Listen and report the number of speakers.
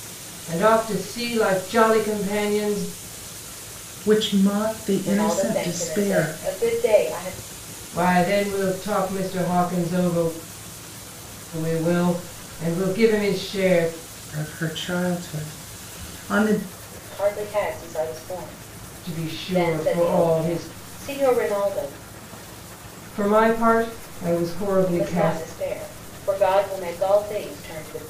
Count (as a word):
three